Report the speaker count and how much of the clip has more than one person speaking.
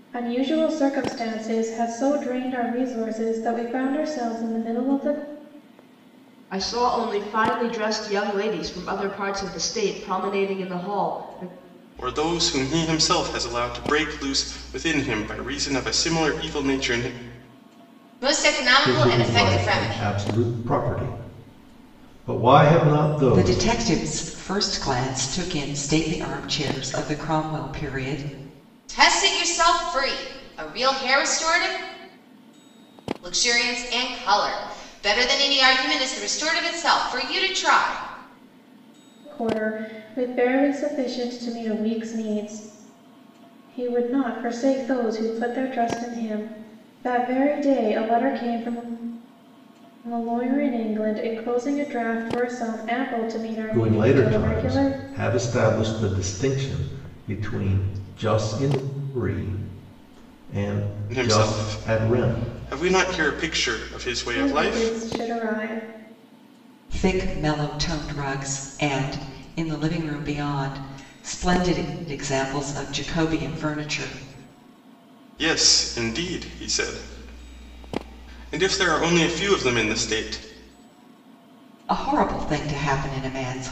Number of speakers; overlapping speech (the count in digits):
6, about 6%